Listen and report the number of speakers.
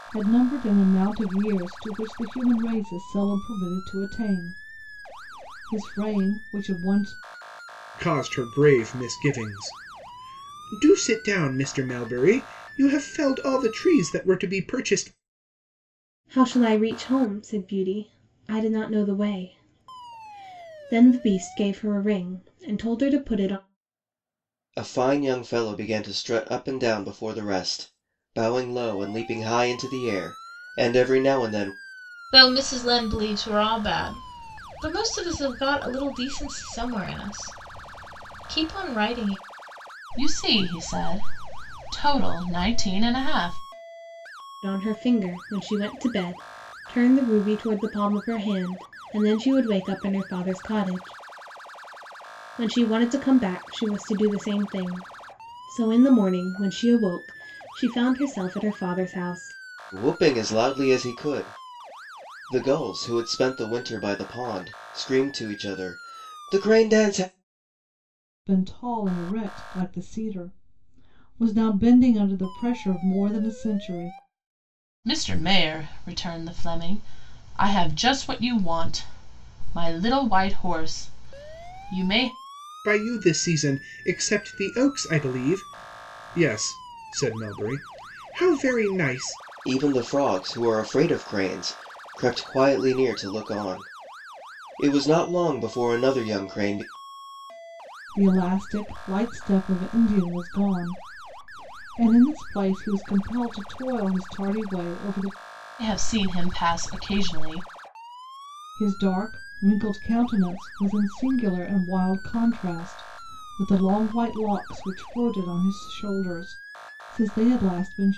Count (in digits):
6